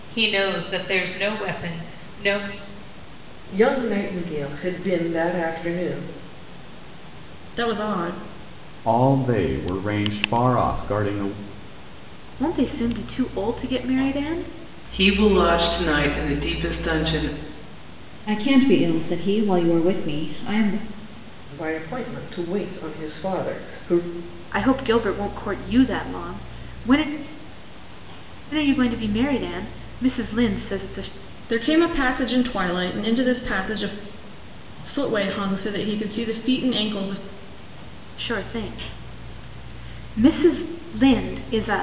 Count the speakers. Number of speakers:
seven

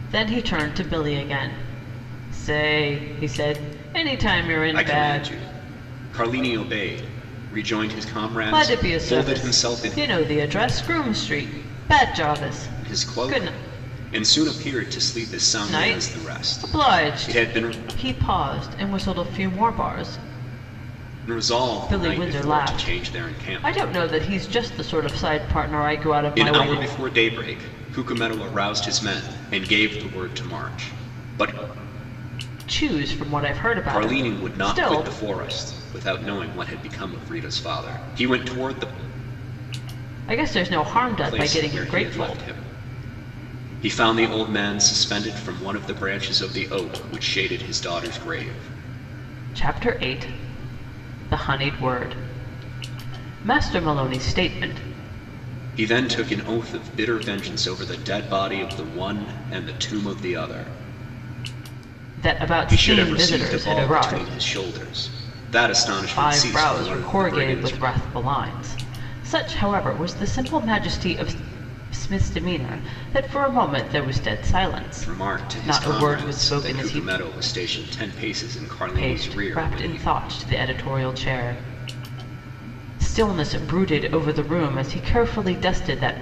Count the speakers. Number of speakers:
two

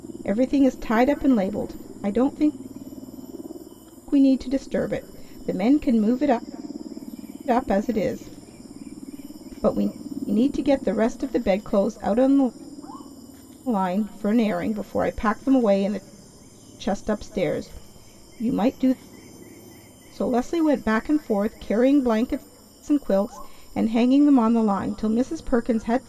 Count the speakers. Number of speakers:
one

